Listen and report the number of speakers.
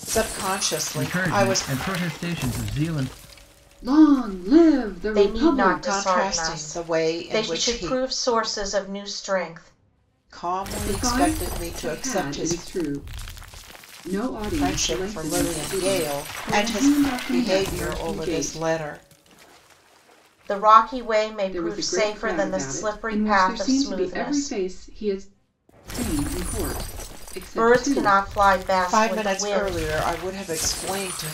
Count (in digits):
4